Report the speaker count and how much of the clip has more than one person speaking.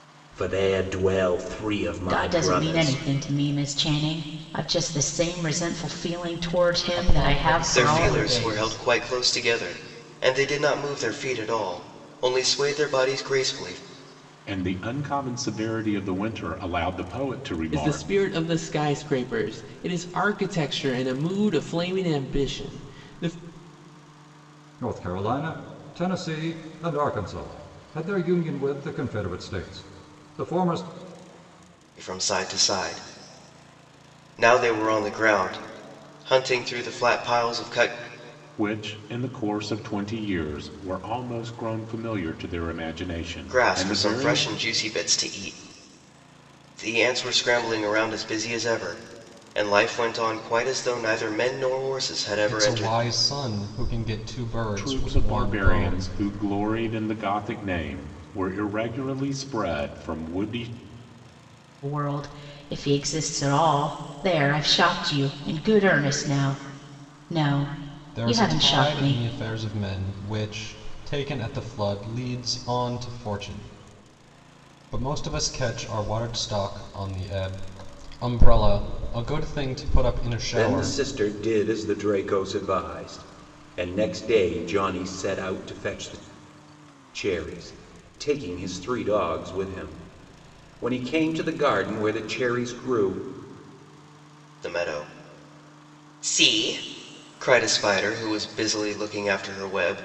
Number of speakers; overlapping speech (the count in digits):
7, about 8%